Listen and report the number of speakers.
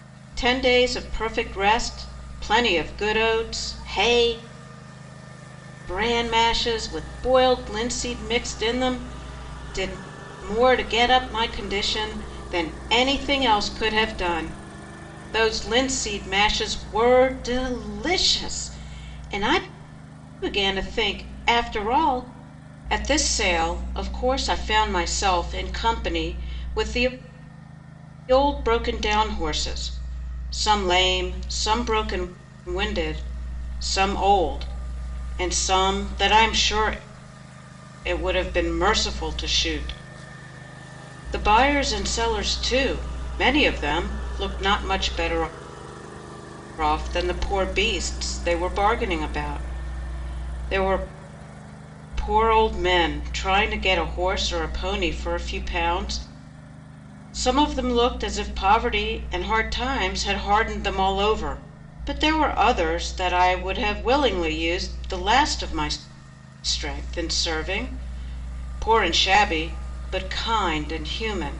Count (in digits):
1